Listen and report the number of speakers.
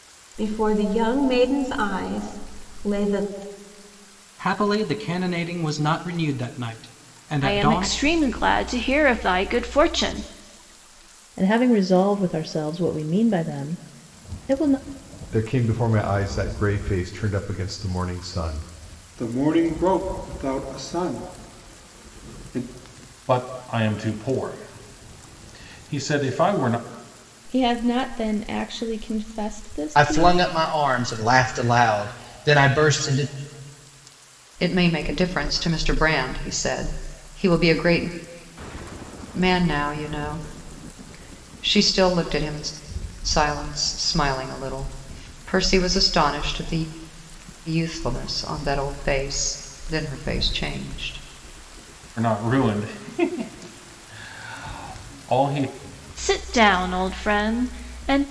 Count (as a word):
ten